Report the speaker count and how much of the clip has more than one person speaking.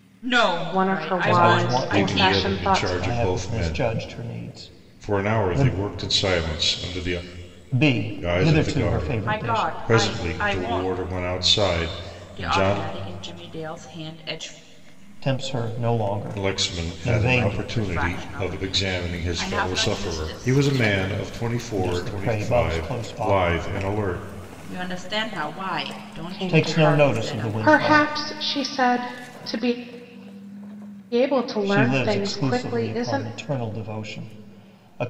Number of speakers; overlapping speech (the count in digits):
4, about 49%